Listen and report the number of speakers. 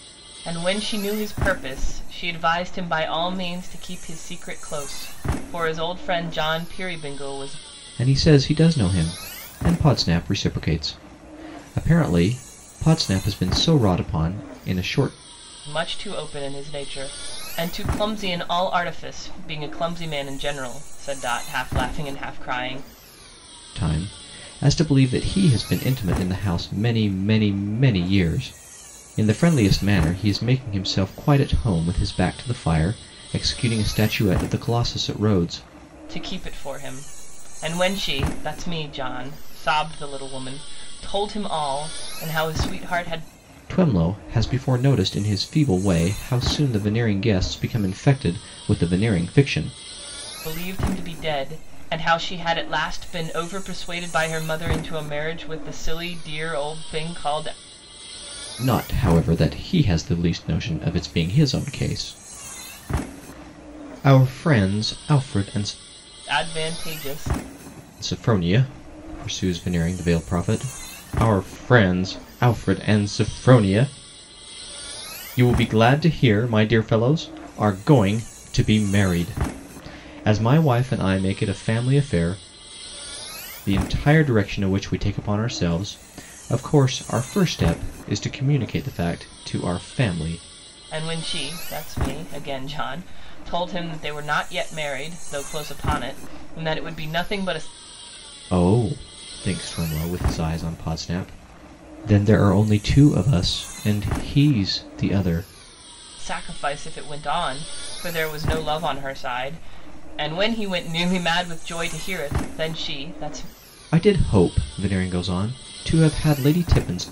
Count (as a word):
two